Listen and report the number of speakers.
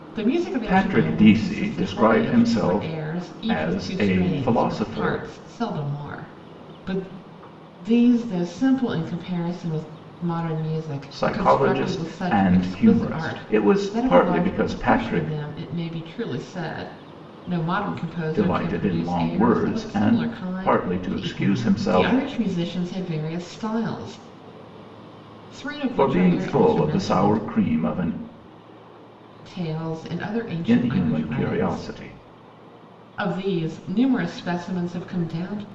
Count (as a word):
two